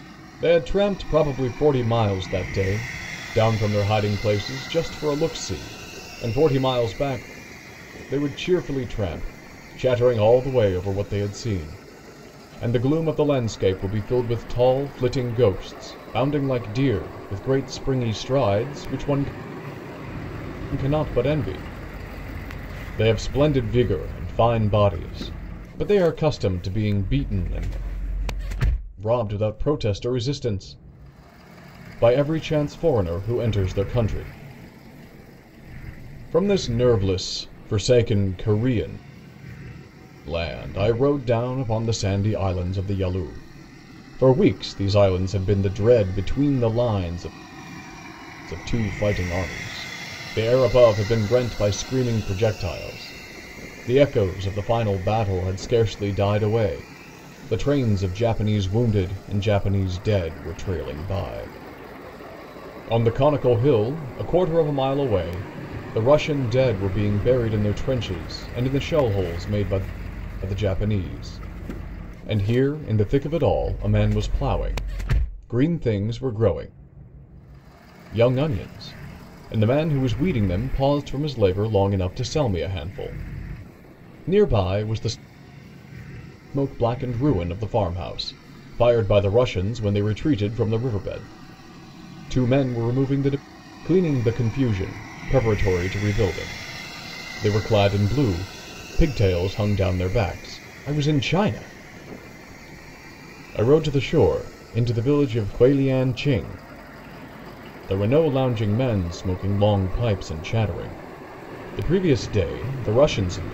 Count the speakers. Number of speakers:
1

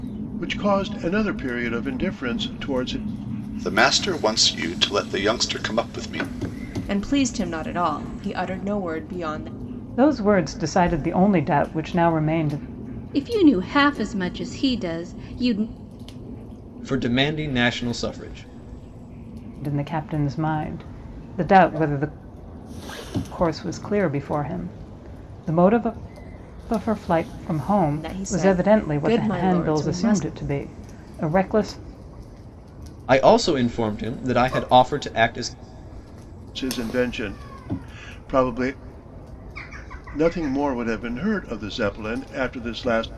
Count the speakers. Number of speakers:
6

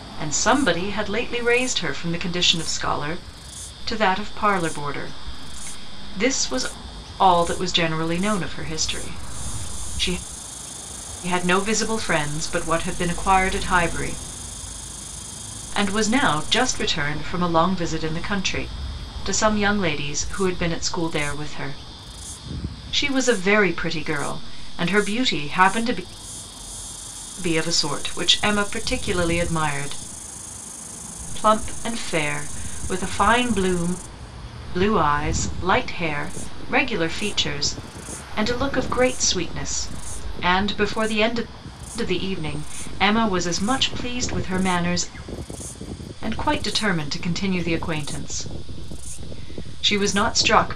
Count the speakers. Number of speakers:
1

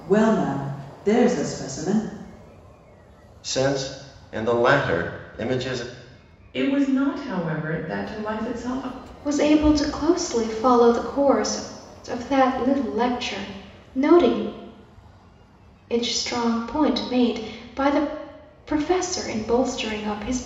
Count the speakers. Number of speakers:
4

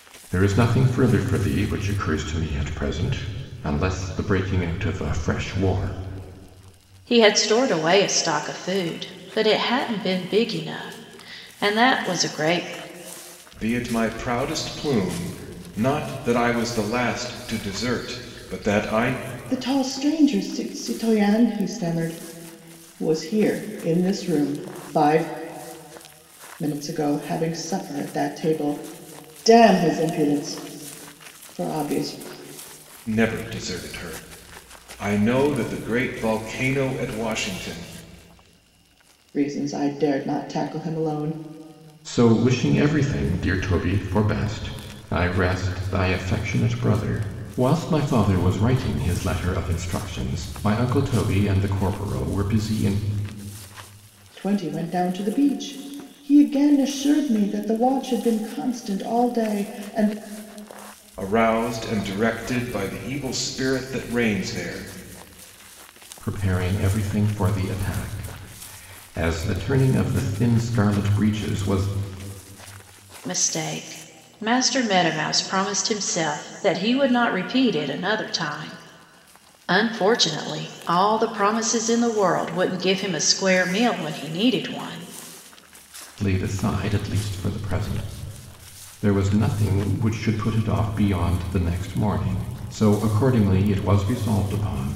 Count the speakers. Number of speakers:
4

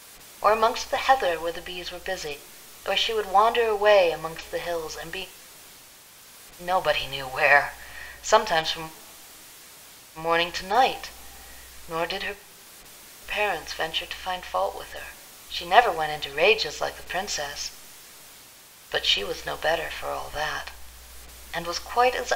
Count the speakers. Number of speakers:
1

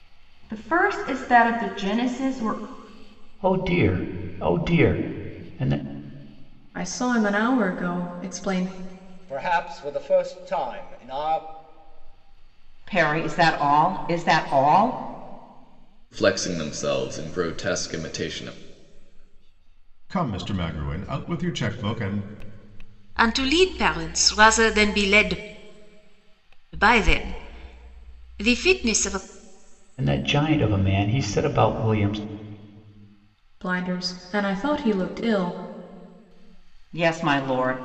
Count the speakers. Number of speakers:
8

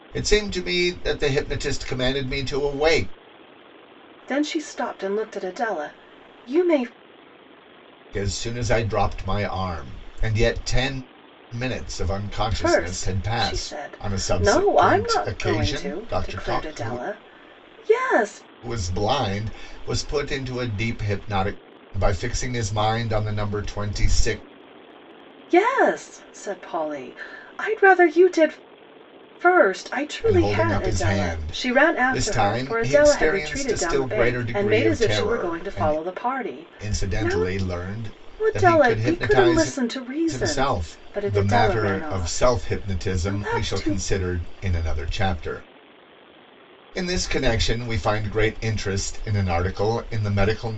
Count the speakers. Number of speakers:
2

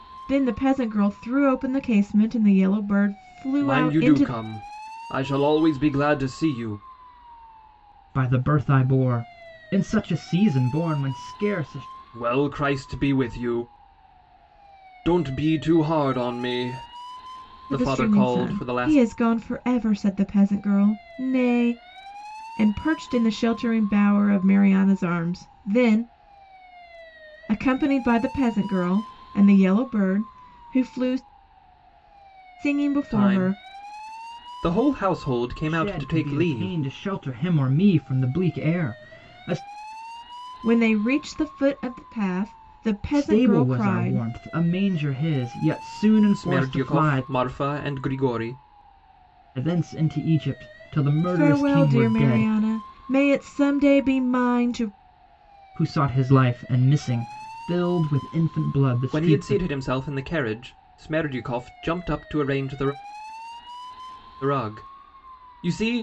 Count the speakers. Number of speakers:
3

